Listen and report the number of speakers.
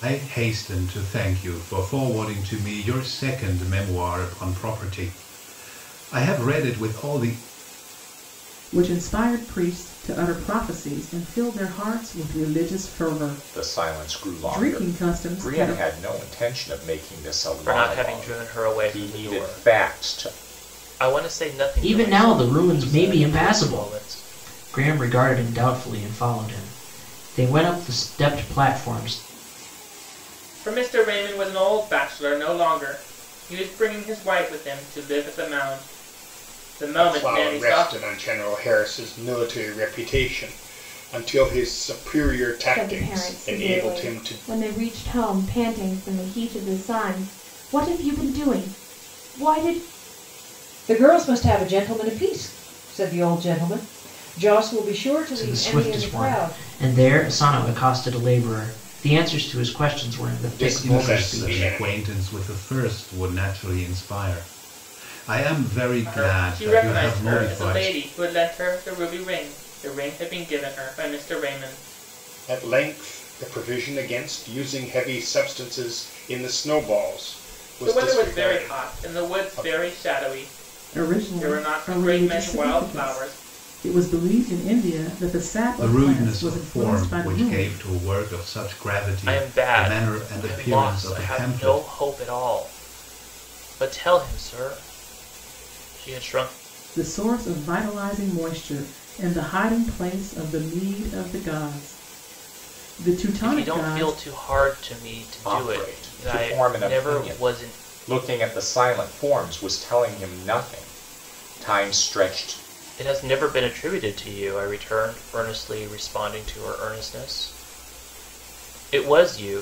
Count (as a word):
nine